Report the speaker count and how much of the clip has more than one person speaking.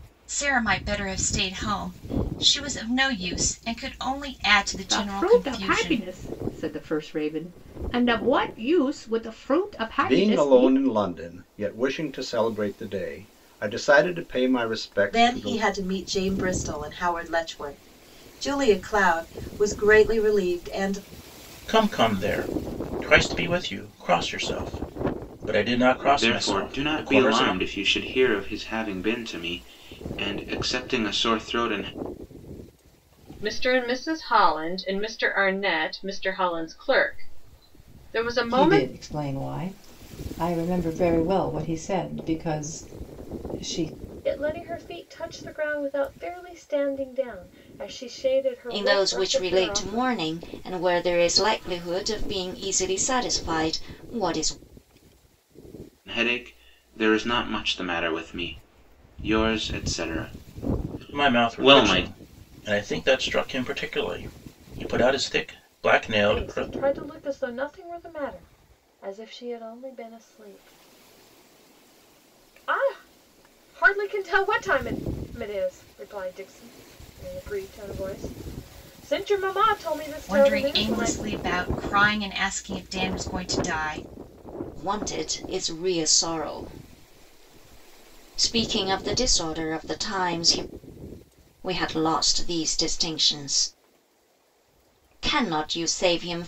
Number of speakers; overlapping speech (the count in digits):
10, about 9%